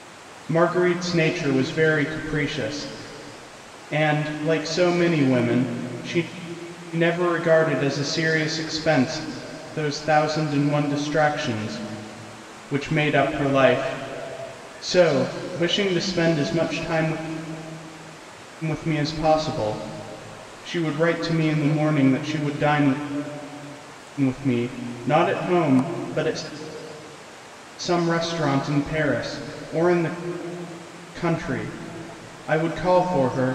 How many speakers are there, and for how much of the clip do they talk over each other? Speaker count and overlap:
one, no overlap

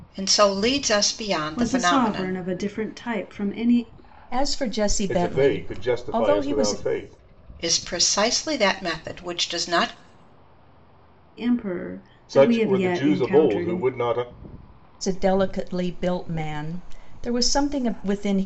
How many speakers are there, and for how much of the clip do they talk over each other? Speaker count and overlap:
four, about 23%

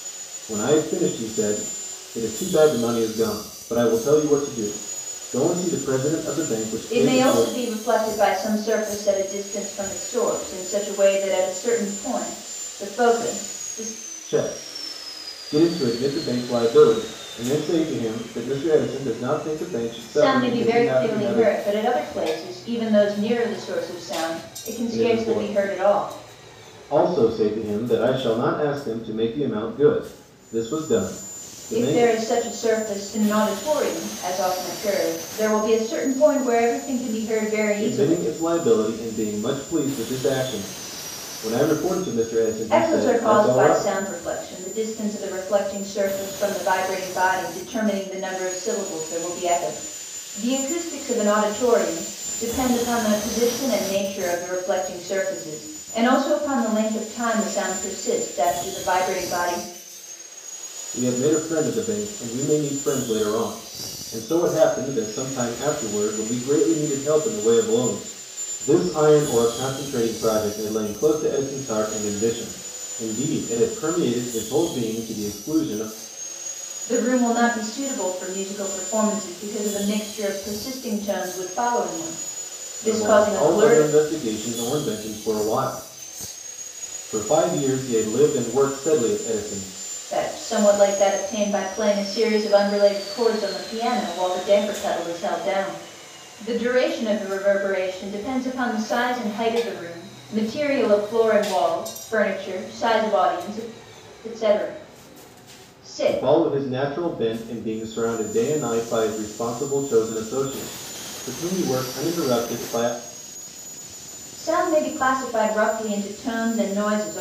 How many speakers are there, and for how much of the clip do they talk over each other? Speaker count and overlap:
two, about 6%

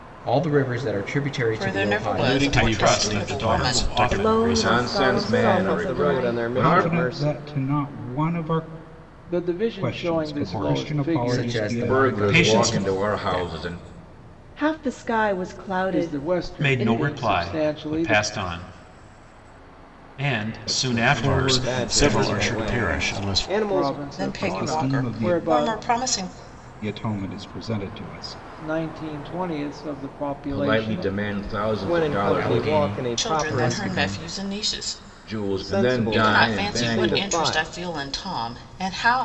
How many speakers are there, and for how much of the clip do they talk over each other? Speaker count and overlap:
nine, about 57%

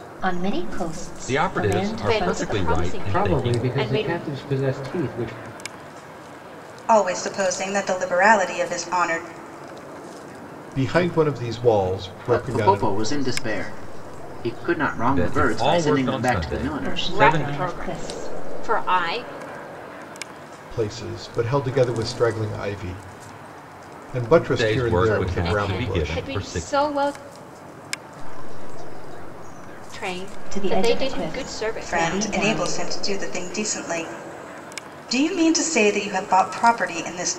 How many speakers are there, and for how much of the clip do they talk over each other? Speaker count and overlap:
eight, about 38%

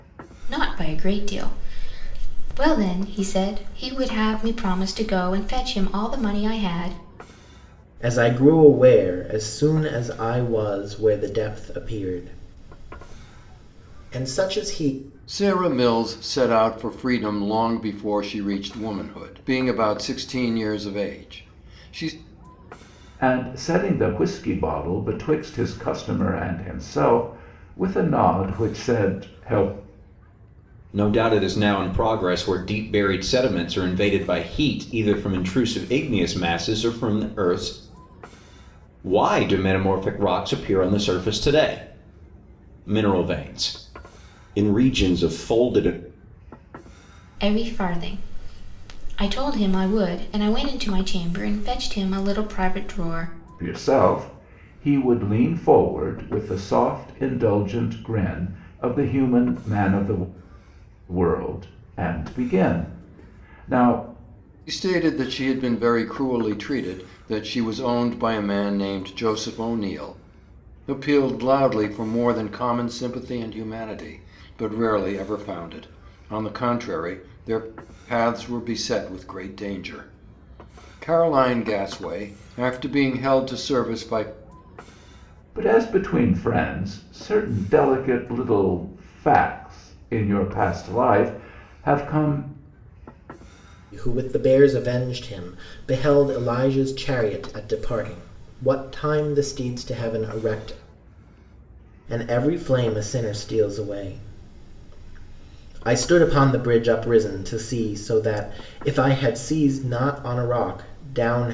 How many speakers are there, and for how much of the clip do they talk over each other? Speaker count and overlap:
five, no overlap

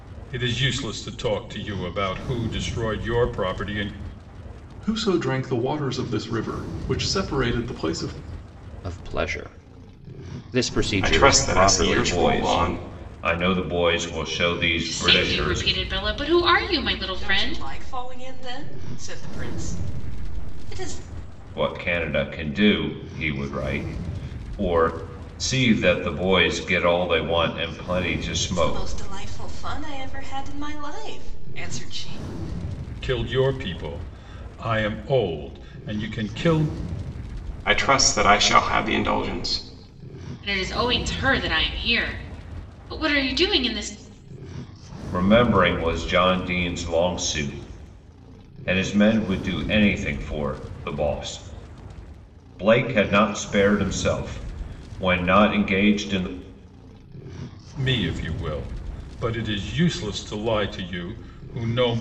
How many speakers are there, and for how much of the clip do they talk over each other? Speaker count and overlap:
seven, about 6%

